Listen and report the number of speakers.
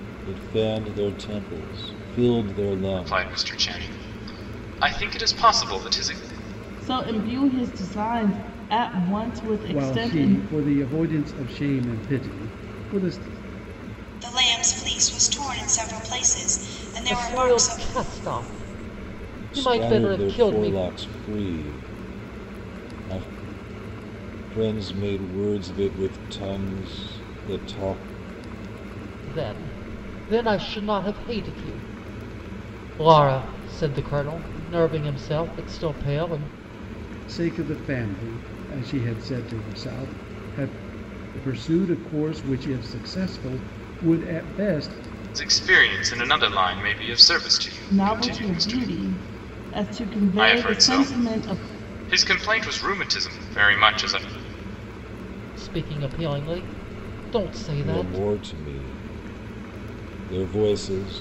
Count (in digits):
6